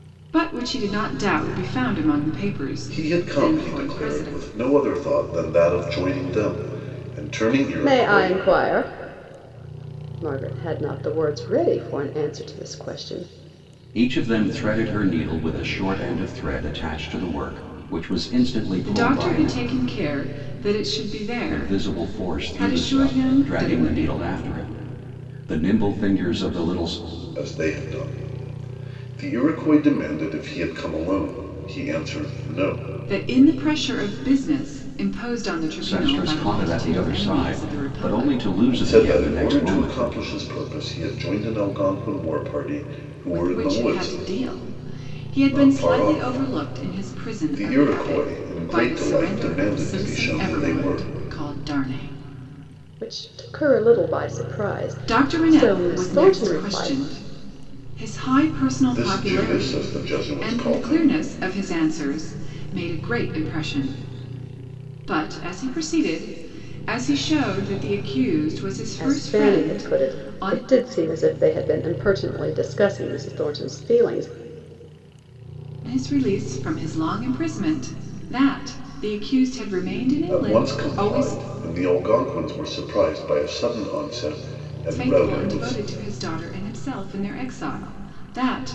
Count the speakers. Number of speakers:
4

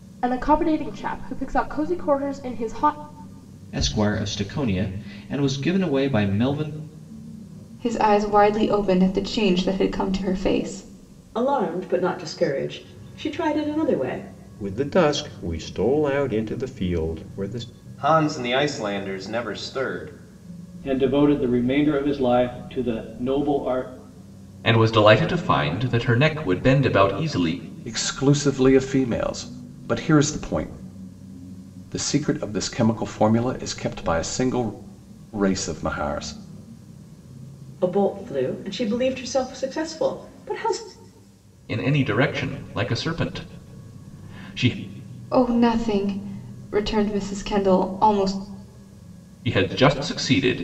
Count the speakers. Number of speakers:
9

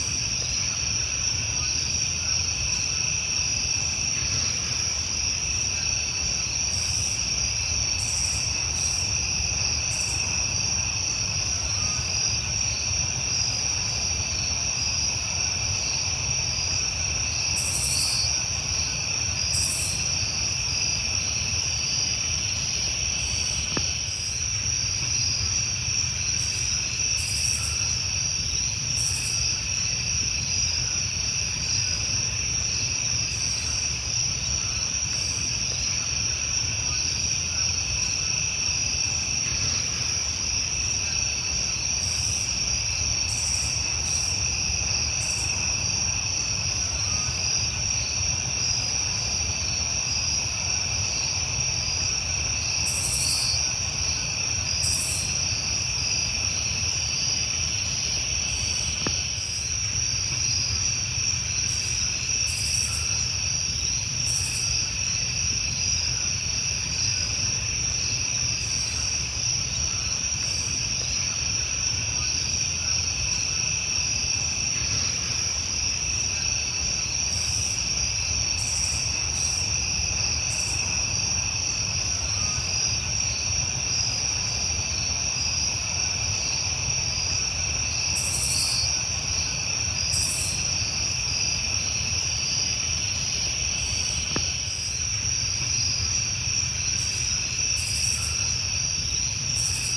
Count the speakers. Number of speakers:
0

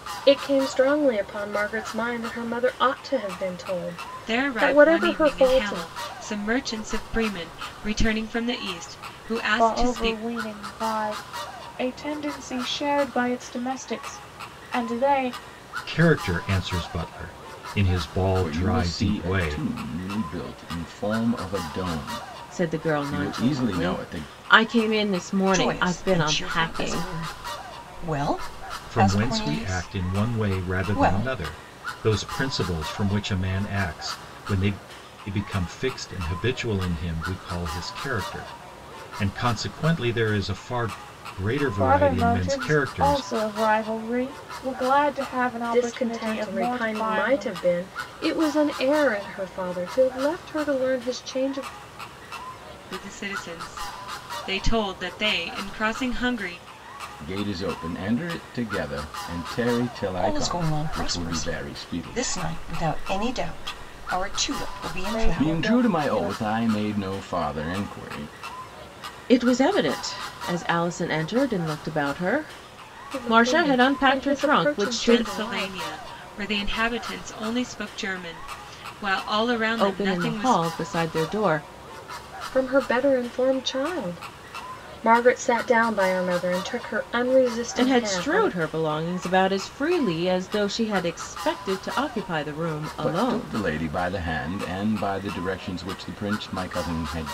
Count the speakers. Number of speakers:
7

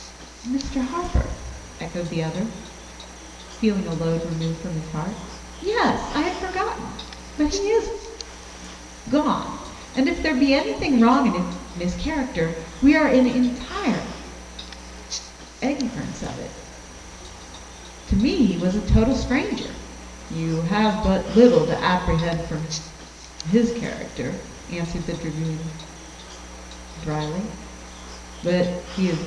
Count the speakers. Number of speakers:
1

